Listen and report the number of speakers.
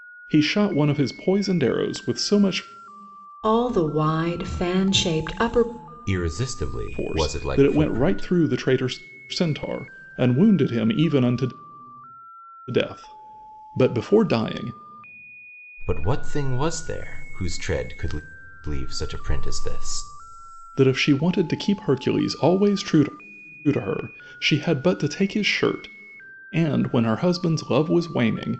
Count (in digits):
3